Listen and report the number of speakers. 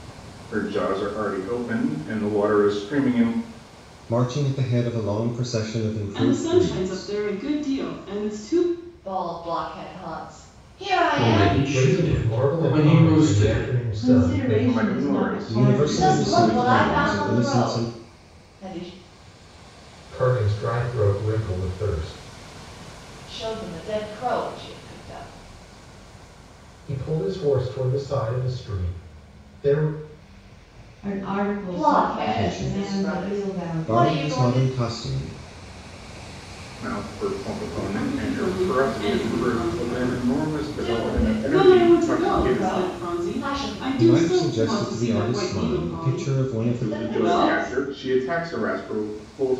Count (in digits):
7